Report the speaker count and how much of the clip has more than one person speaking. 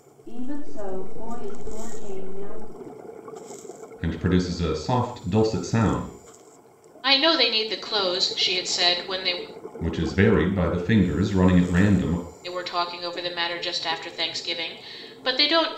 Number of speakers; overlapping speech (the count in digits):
3, no overlap